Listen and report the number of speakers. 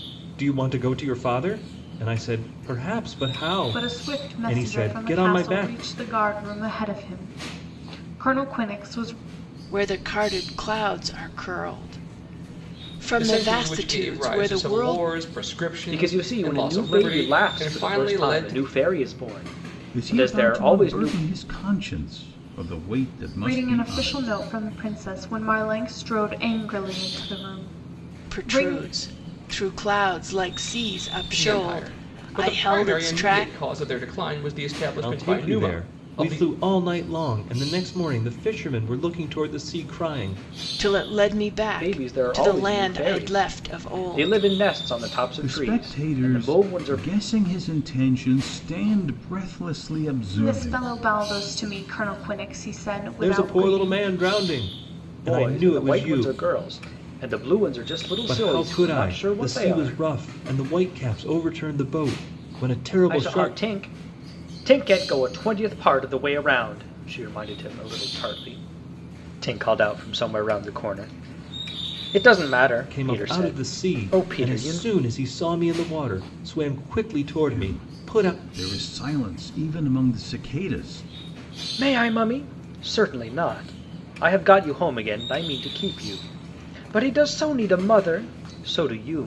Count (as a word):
six